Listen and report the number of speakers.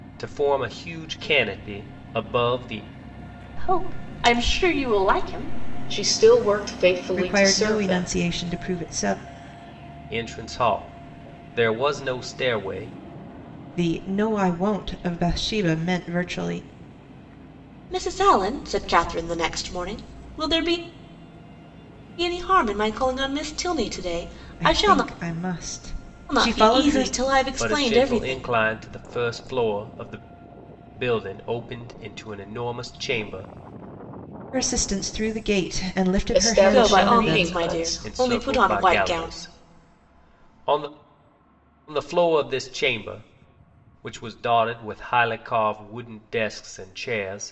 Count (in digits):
4